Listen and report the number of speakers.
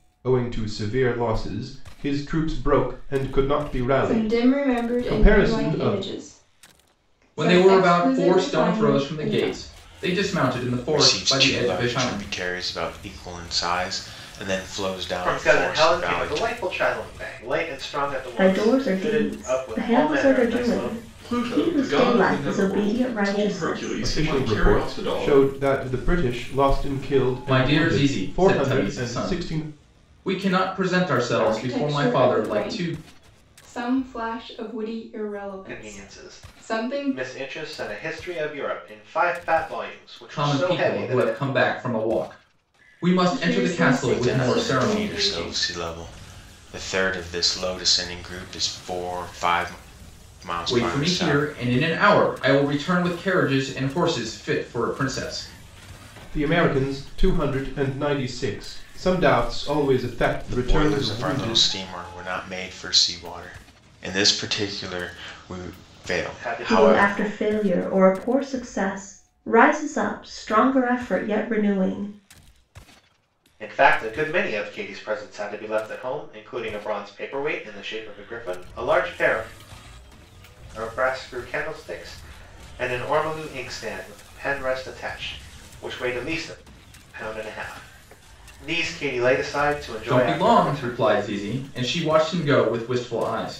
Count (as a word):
seven